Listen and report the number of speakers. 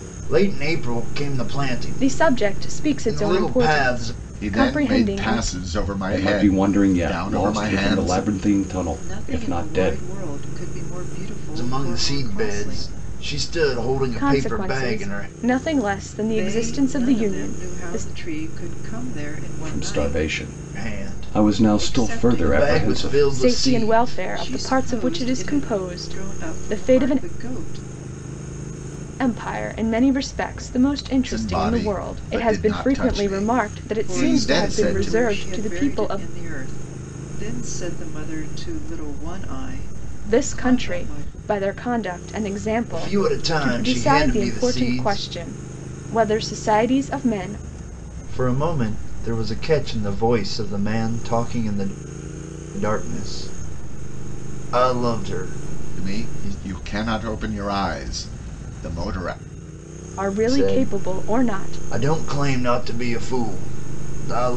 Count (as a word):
five